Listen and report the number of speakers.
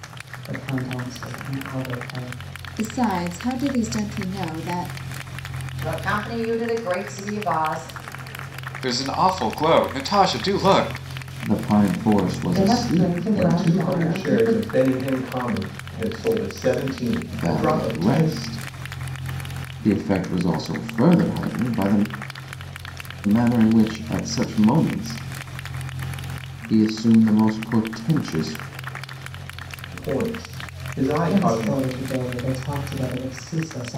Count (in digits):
7